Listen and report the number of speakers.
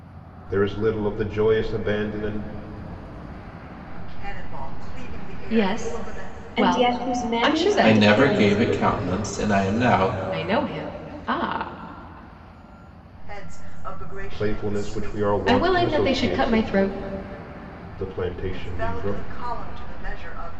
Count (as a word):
five